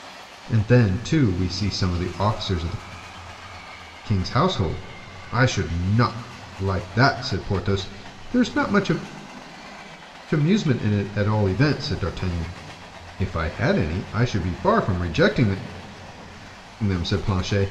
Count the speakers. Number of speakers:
one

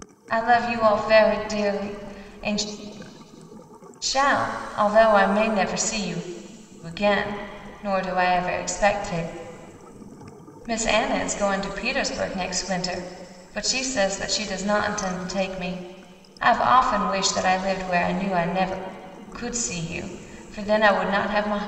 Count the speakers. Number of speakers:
one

